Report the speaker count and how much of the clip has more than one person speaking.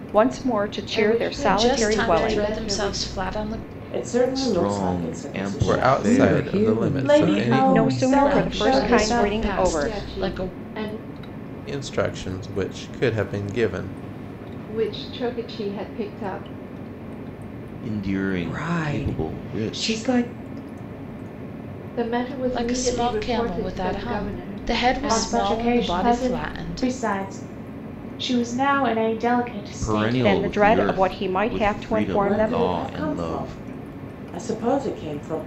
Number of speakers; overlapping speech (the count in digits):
8, about 51%